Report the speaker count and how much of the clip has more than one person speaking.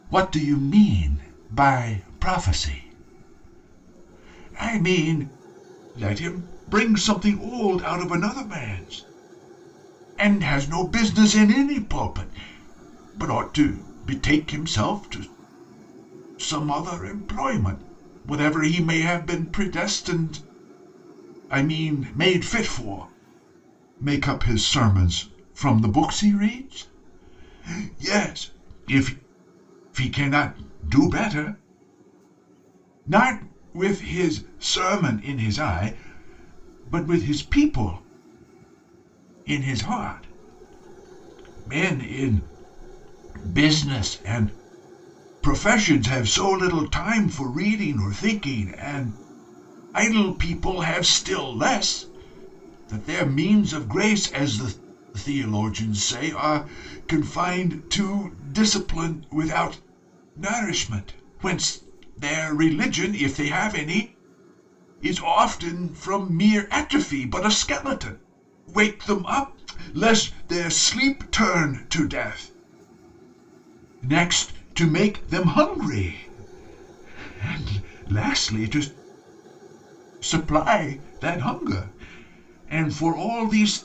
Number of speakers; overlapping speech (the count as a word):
one, no overlap